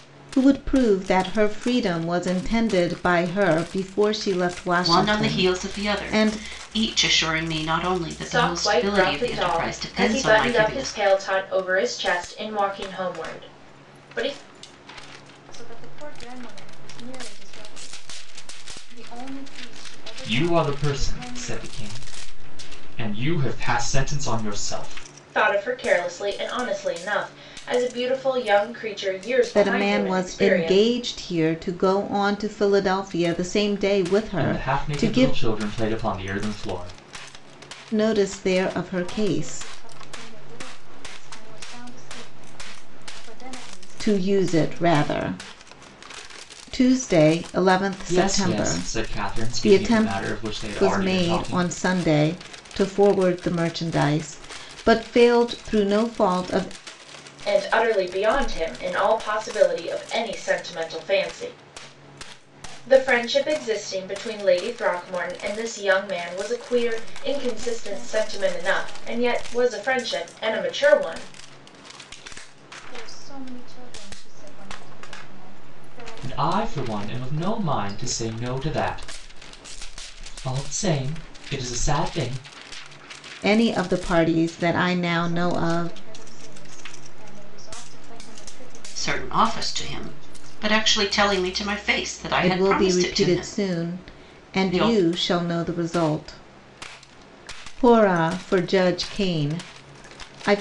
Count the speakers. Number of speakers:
5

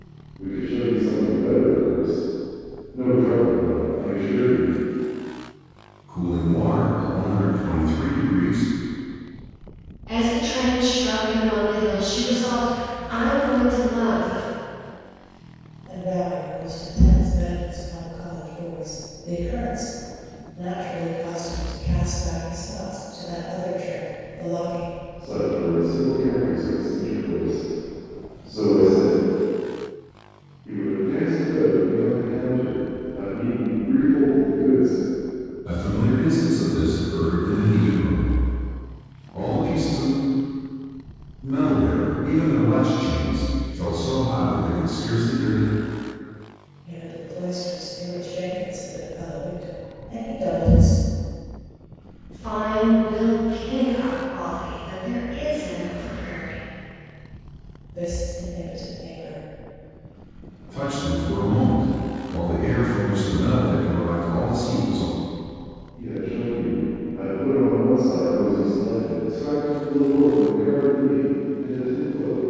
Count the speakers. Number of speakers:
4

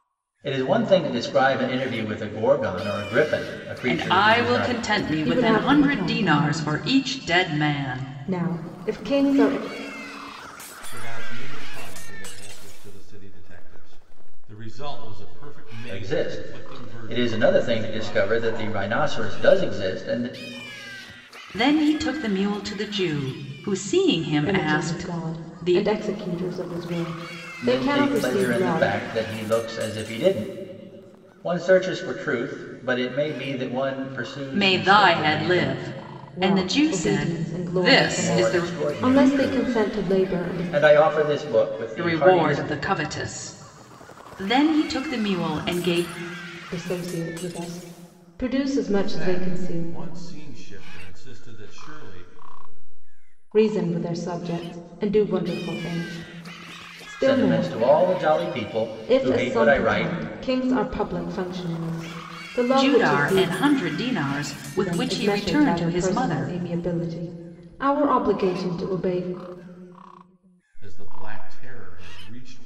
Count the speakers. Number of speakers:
4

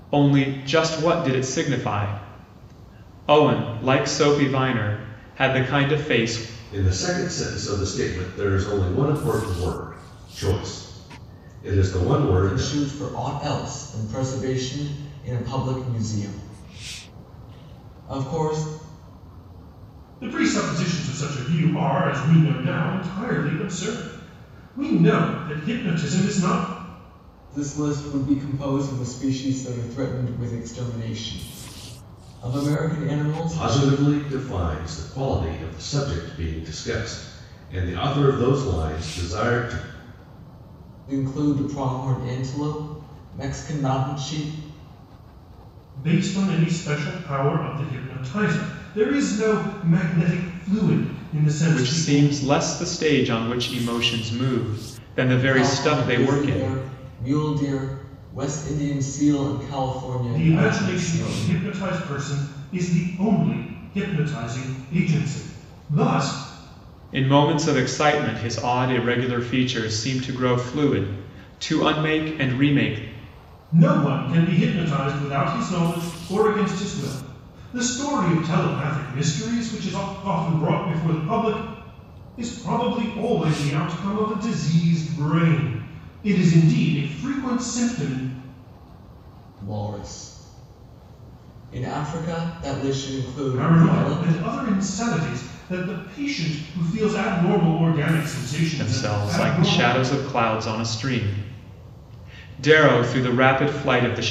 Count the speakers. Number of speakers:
4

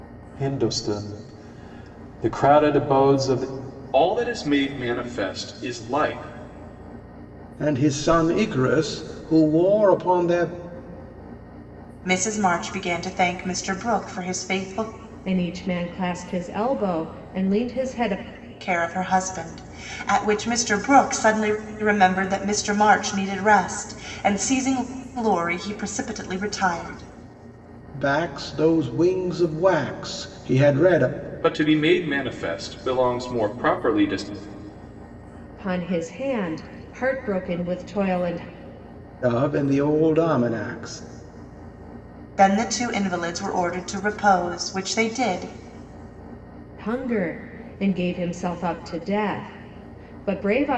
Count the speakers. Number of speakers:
5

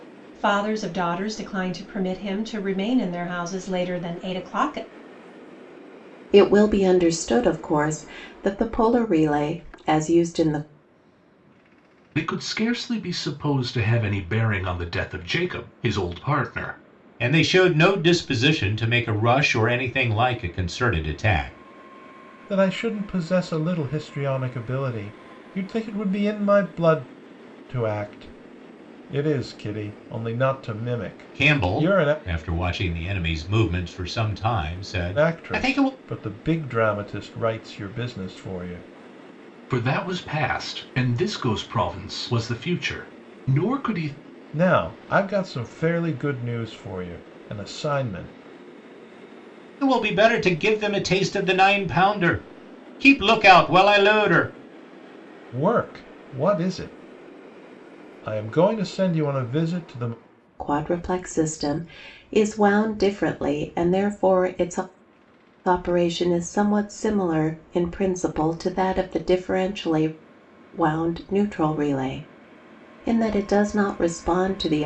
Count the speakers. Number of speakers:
5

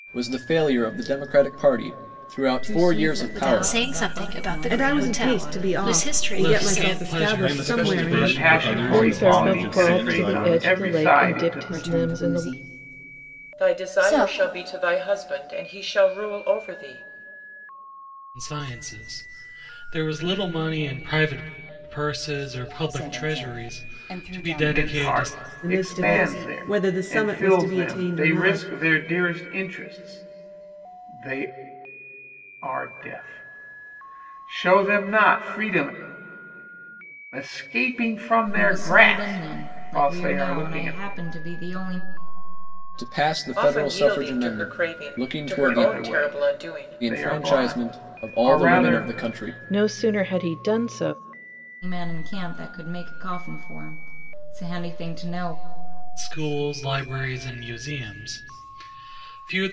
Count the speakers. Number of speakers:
10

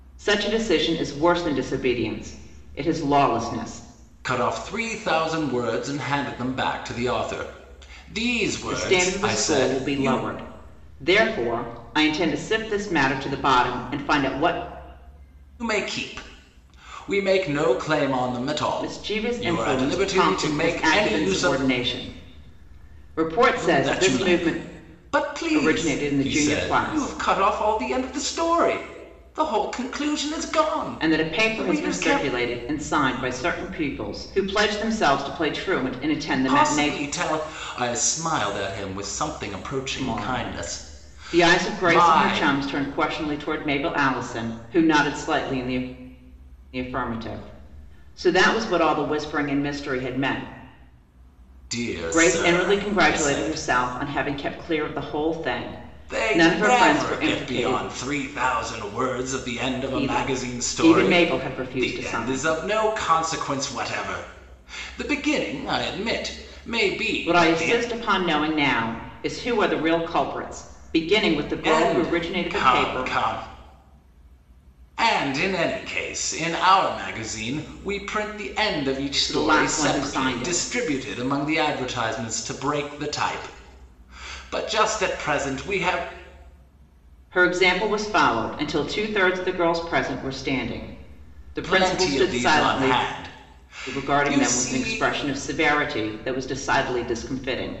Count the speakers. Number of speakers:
2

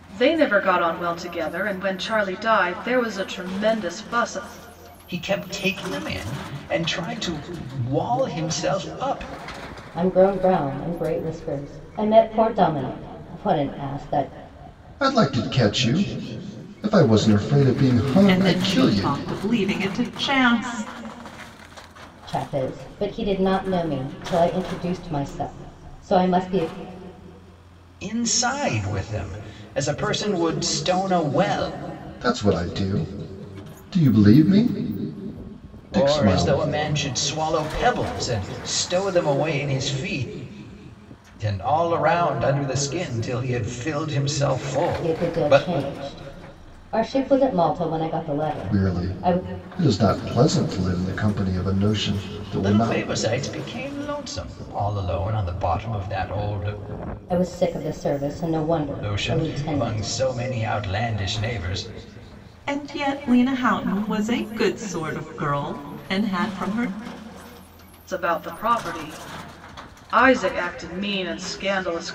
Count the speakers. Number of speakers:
5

